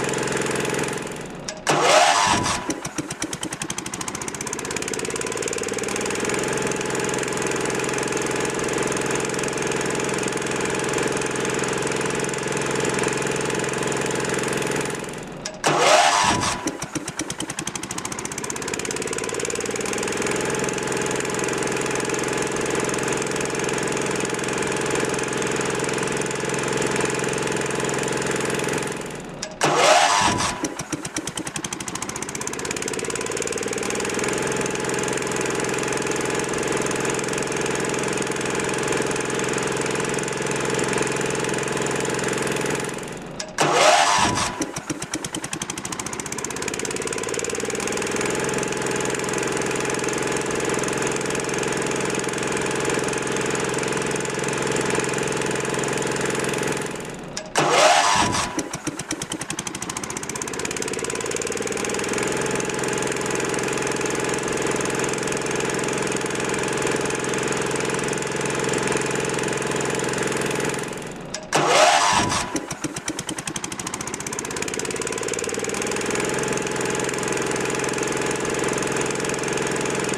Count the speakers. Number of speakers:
zero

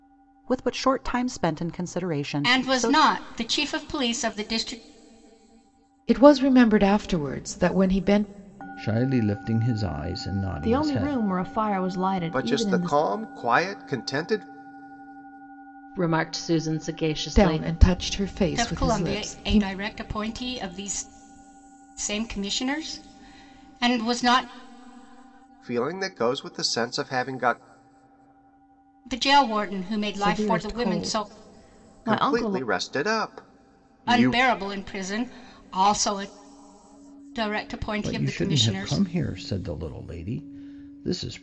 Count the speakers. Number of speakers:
seven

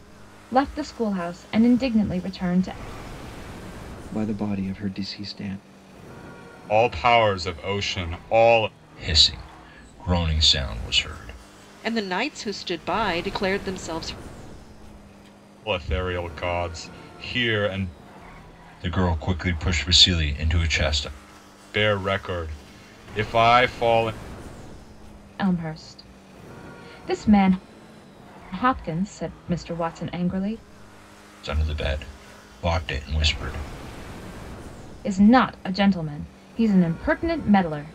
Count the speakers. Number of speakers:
five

